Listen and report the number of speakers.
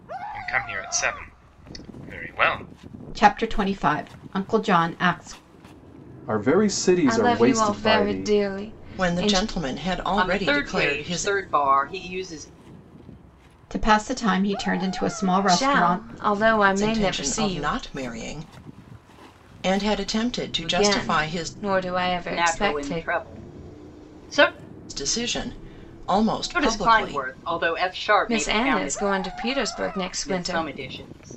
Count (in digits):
6